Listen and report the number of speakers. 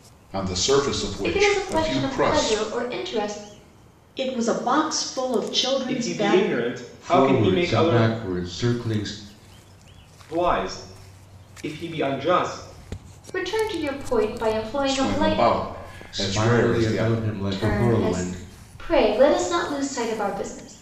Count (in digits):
5